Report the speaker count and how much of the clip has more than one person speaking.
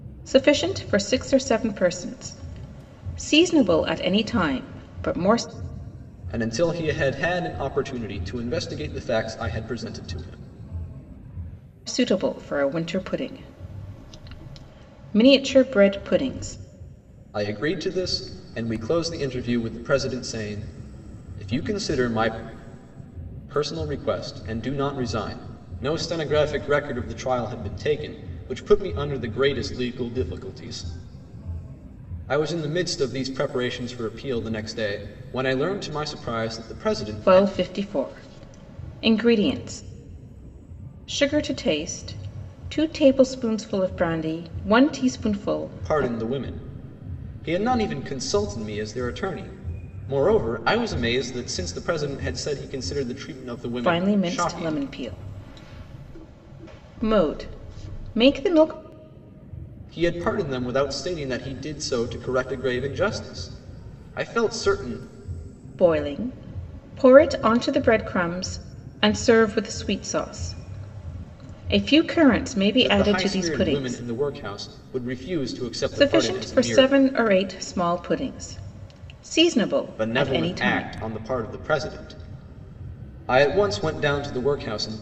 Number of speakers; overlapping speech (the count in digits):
2, about 6%